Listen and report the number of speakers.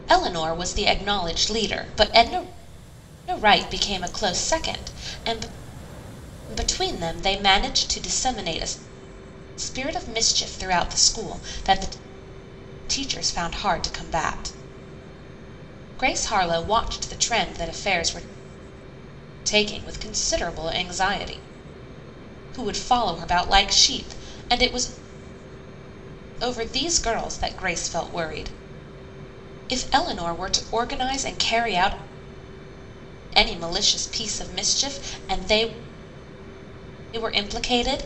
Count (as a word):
one